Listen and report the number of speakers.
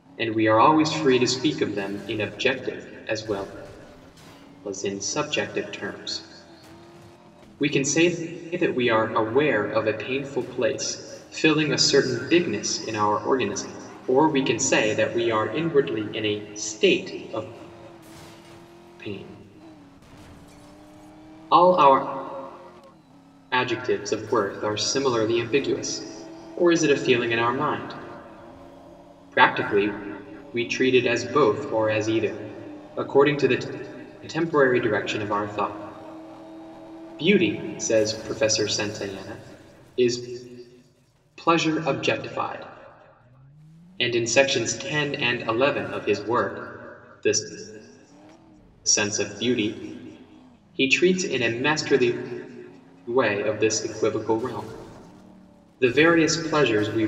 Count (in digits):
1